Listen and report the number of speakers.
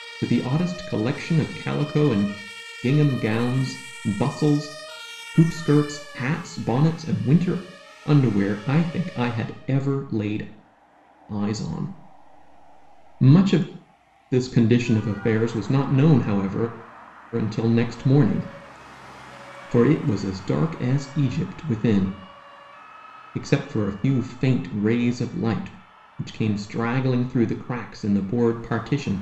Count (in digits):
1